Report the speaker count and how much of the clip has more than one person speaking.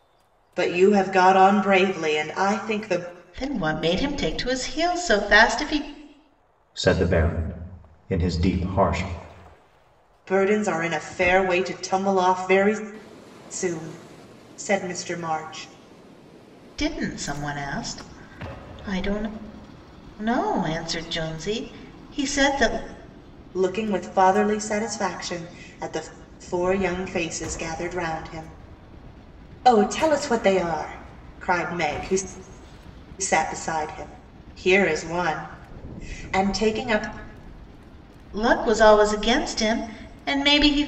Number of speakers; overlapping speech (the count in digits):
3, no overlap